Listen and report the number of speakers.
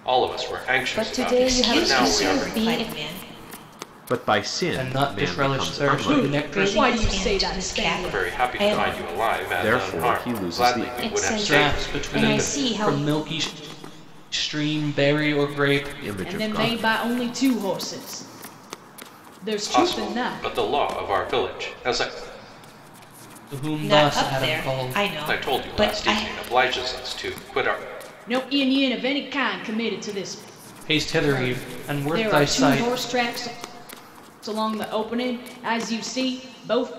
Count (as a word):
six